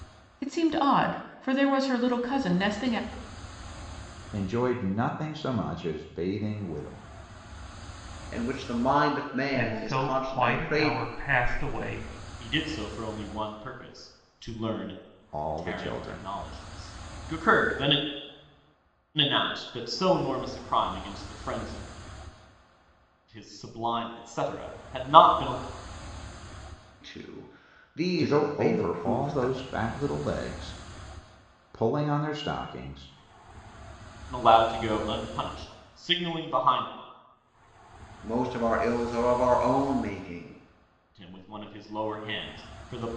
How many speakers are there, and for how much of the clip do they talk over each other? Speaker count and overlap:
five, about 9%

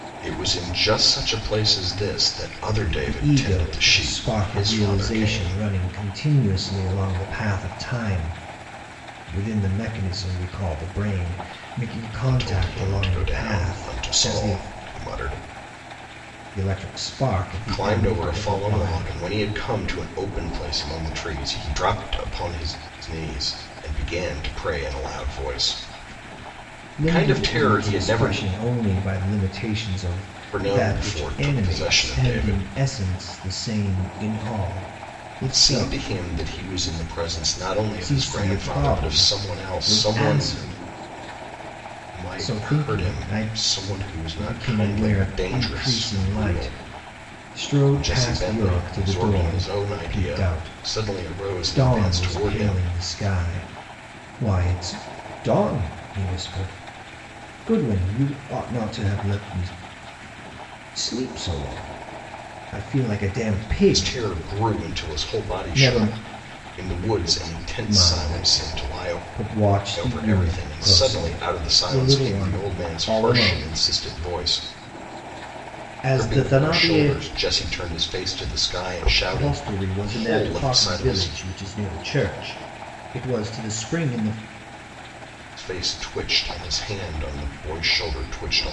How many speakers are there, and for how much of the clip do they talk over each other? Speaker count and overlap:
two, about 37%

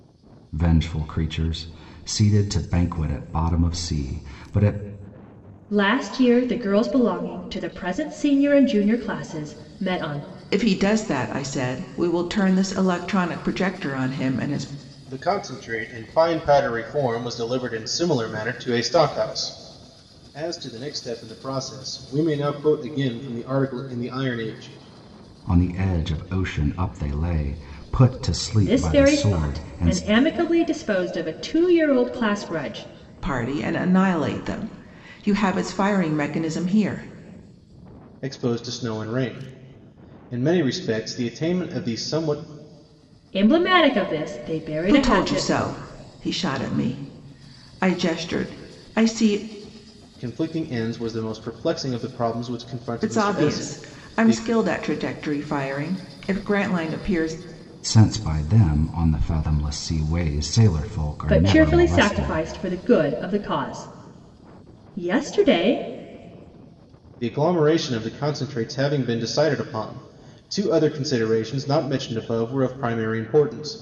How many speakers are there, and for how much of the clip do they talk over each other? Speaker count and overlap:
four, about 6%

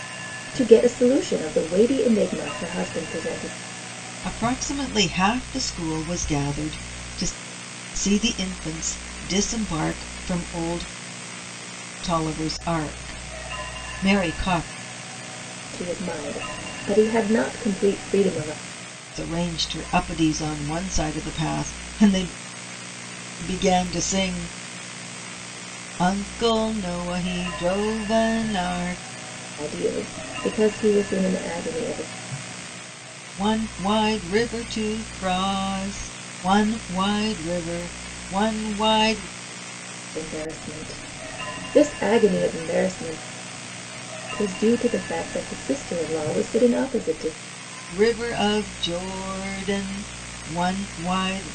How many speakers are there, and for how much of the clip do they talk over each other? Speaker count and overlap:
two, no overlap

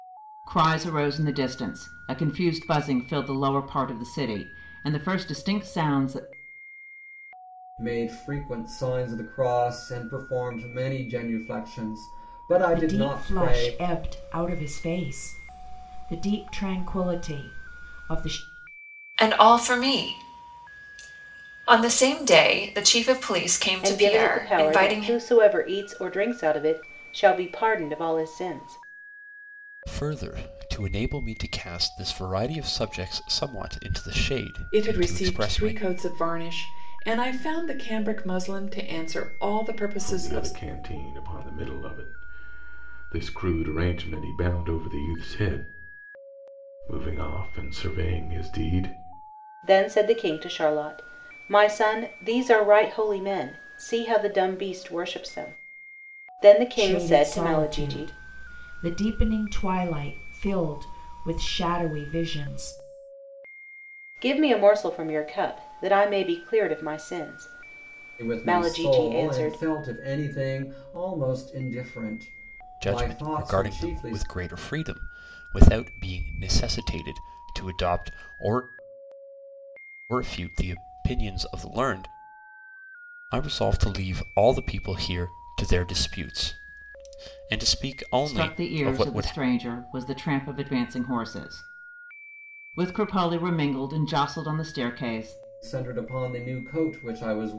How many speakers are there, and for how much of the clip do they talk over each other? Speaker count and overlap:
eight, about 10%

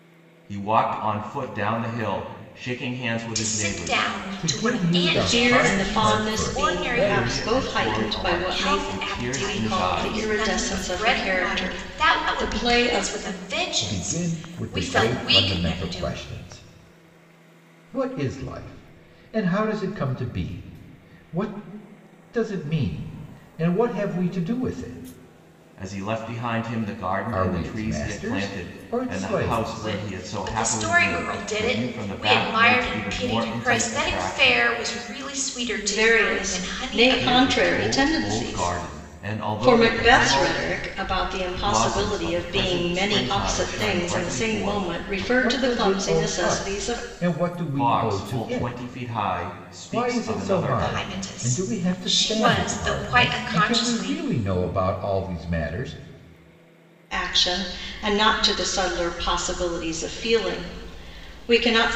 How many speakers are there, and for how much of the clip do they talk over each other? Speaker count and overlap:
four, about 55%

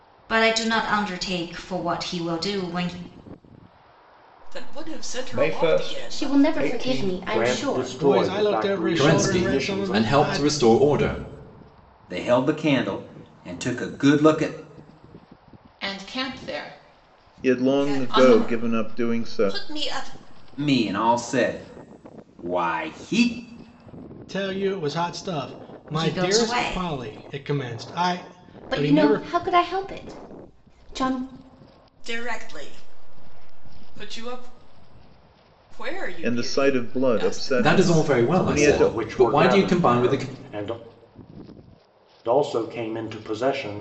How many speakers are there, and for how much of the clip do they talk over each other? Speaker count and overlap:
ten, about 30%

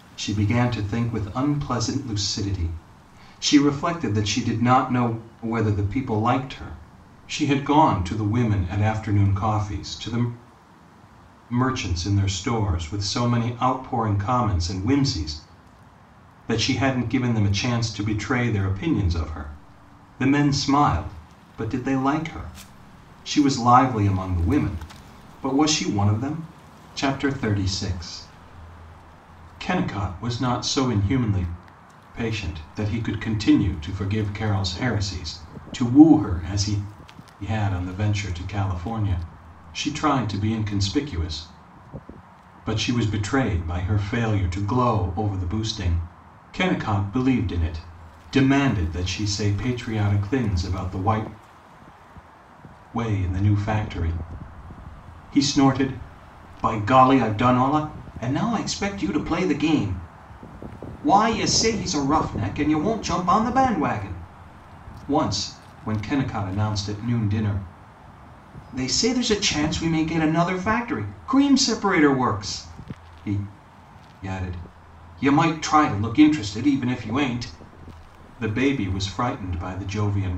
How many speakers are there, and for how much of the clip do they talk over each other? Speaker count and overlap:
one, no overlap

